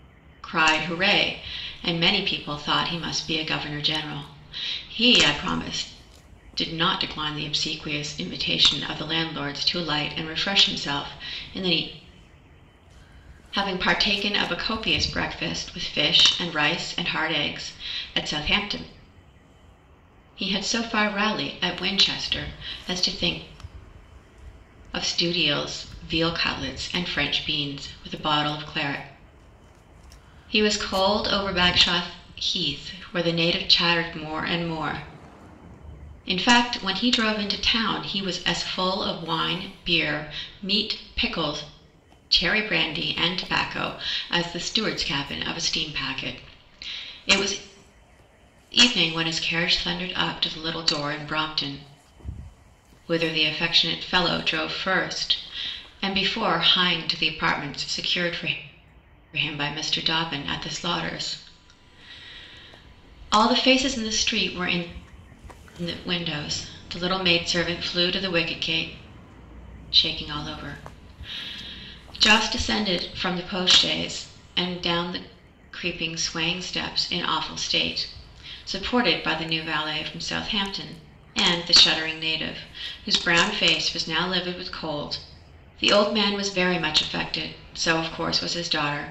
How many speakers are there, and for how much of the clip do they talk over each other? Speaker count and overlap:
one, no overlap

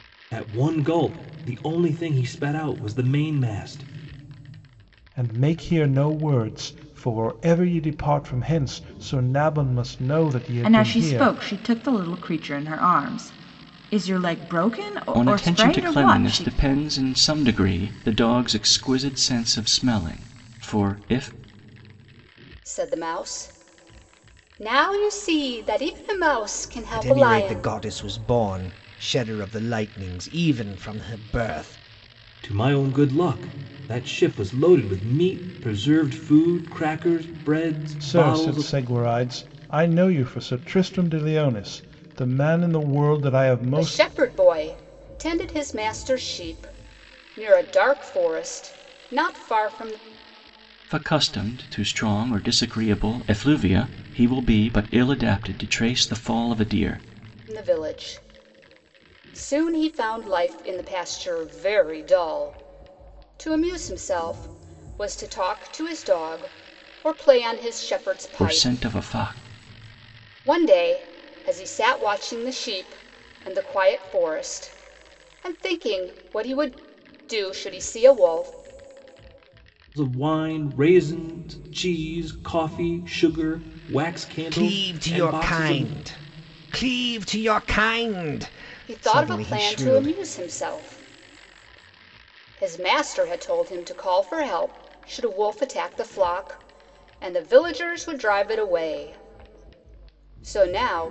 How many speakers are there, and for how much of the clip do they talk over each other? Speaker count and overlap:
six, about 7%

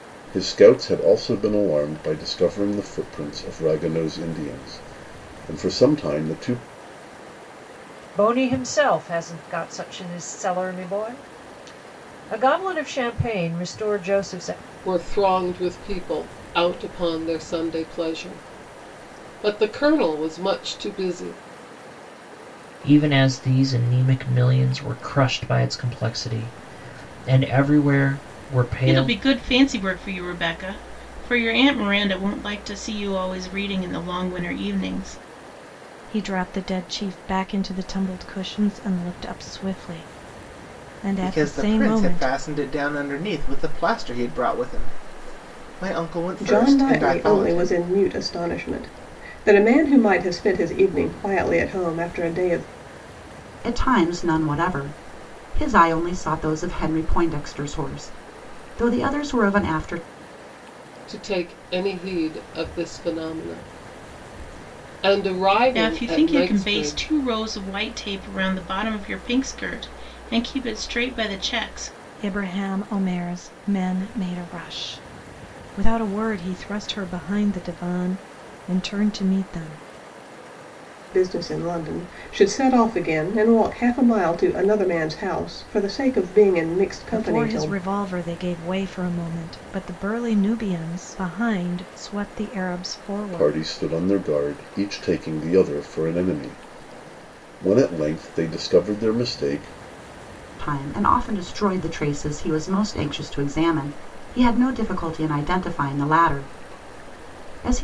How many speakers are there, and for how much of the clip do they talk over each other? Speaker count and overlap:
nine, about 5%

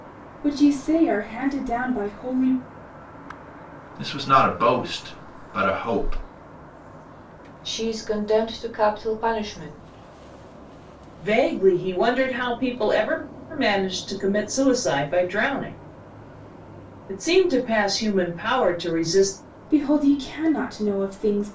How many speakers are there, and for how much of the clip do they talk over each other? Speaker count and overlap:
four, no overlap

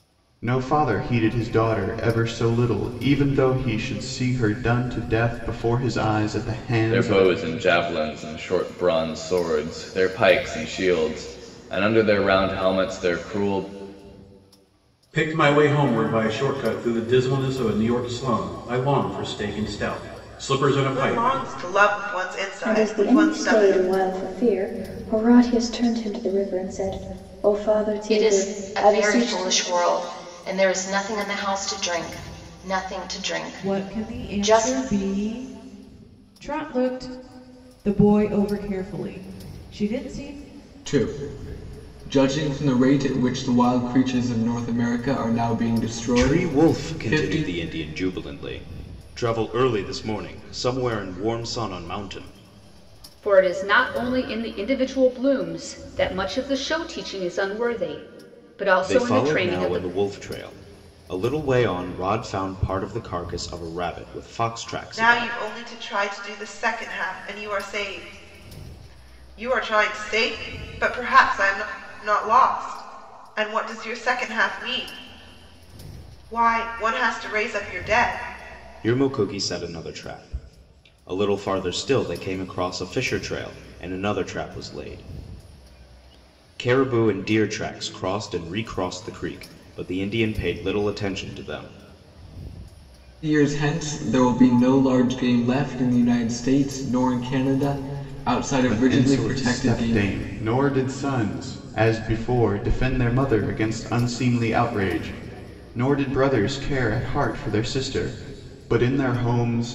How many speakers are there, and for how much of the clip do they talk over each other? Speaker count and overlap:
ten, about 8%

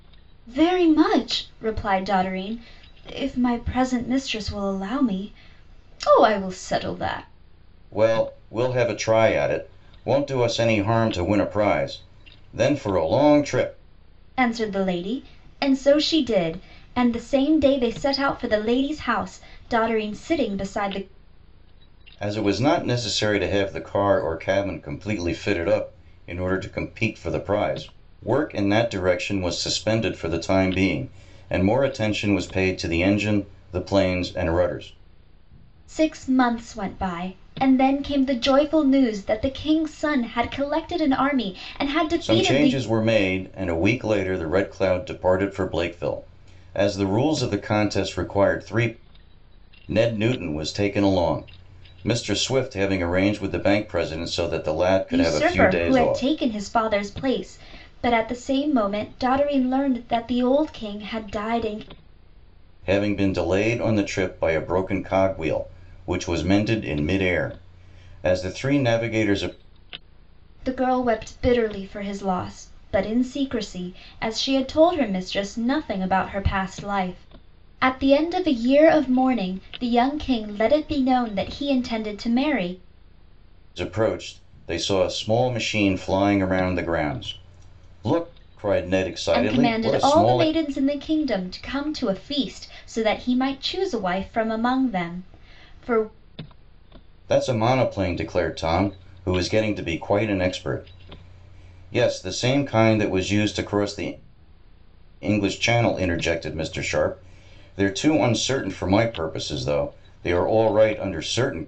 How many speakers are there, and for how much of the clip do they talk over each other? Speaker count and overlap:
two, about 3%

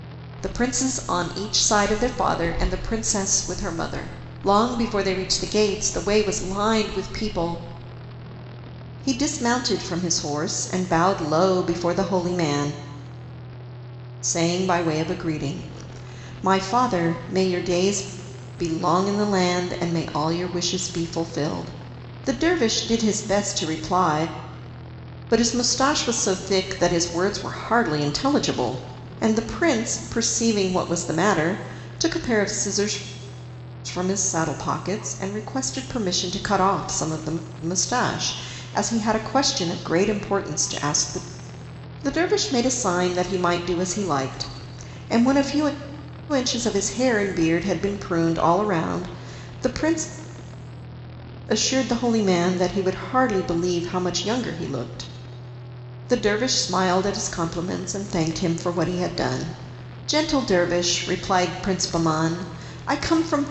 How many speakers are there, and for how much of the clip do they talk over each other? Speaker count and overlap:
one, no overlap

